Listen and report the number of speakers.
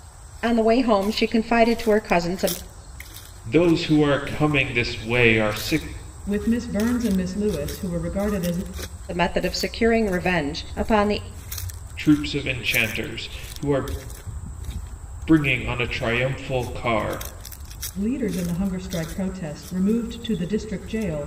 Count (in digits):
3